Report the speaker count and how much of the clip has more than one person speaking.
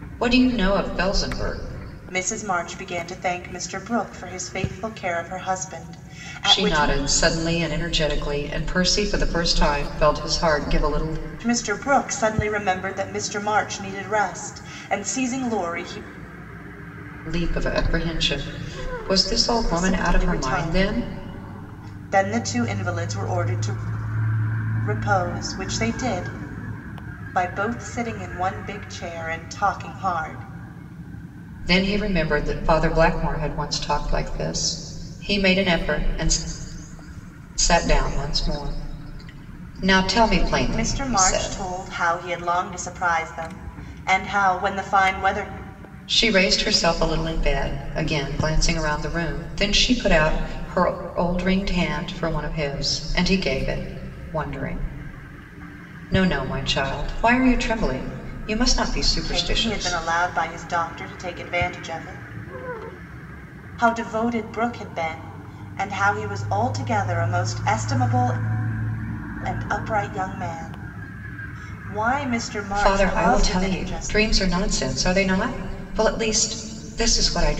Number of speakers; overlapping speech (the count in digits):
2, about 7%